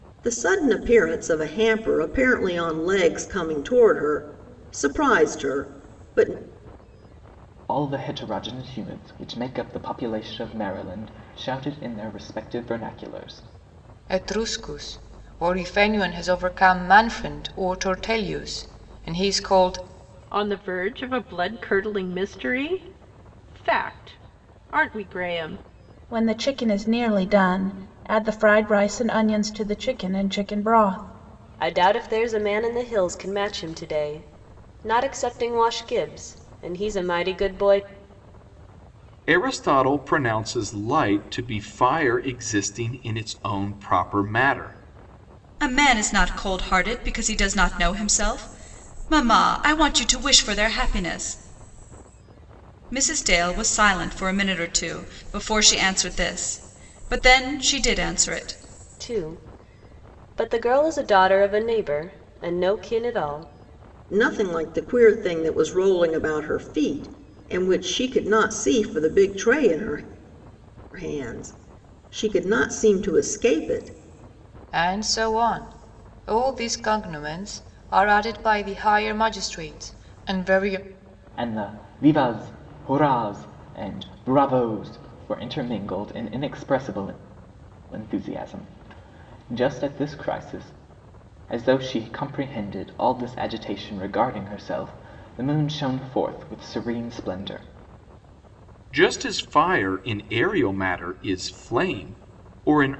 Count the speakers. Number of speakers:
8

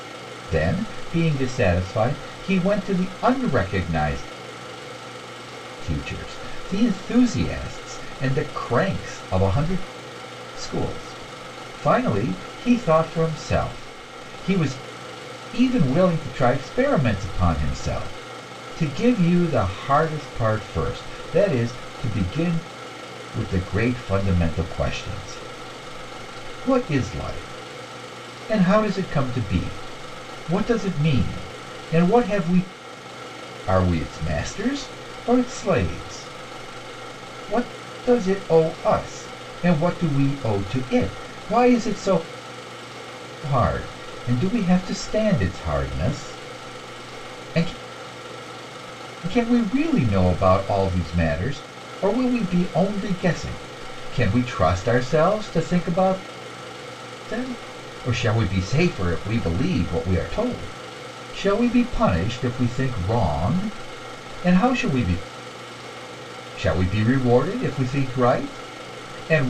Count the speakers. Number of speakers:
1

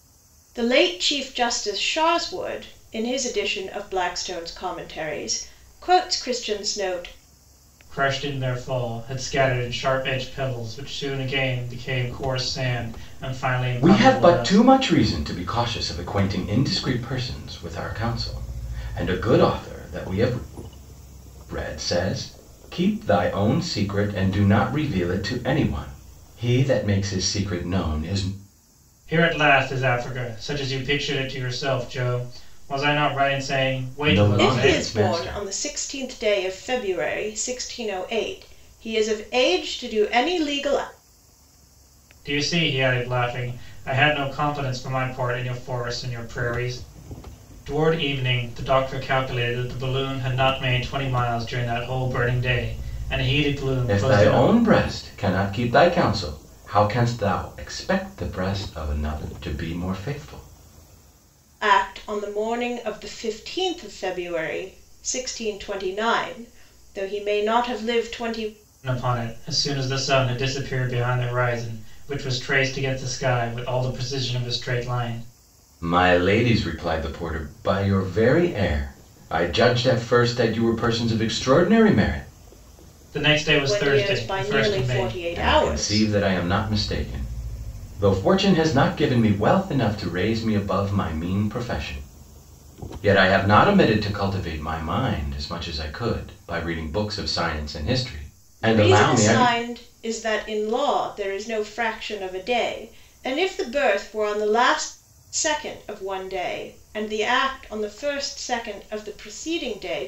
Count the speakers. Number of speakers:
3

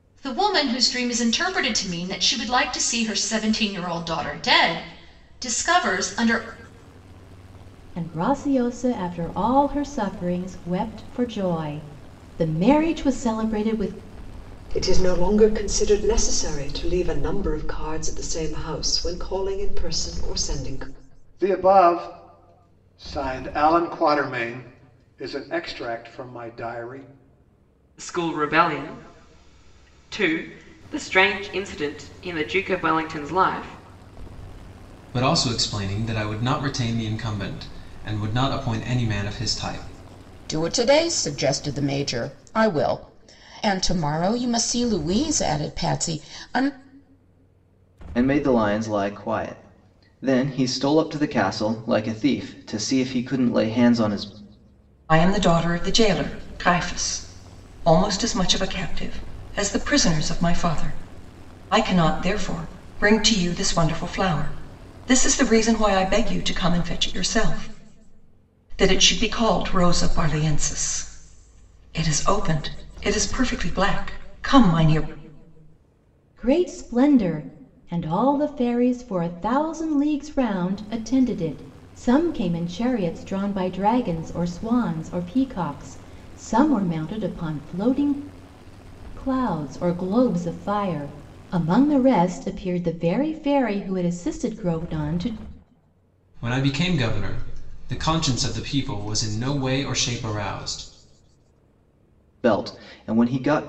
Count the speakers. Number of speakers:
9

